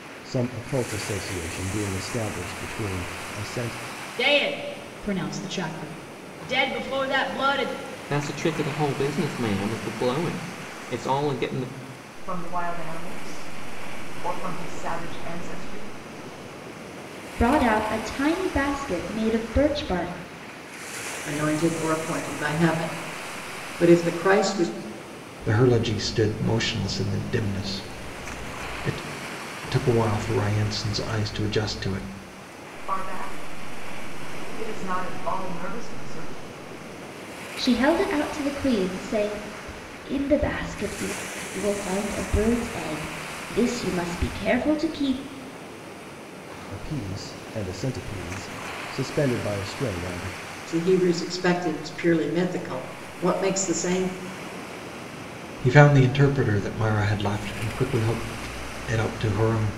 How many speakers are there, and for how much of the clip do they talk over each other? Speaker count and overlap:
seven, no overlap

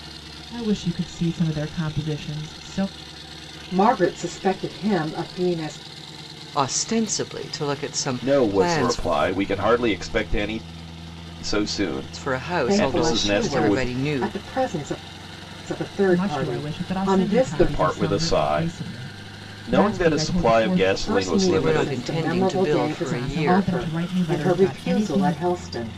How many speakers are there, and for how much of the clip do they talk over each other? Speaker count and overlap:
four, about 44%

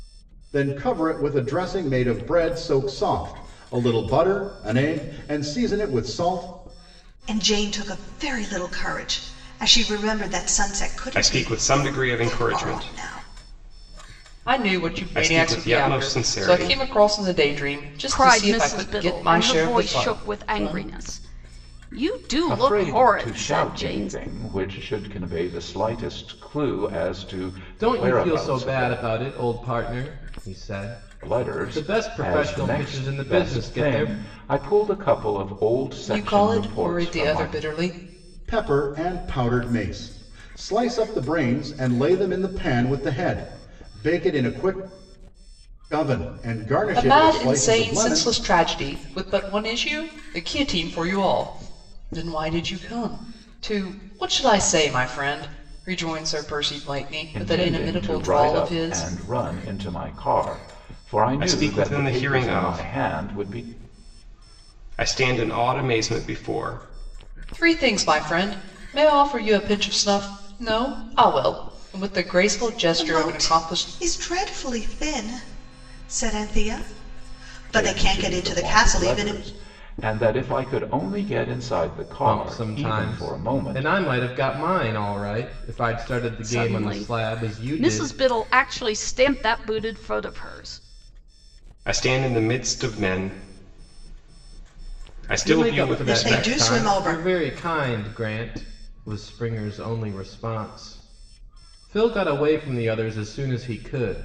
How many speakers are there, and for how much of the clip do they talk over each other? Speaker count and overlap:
seven, about 27%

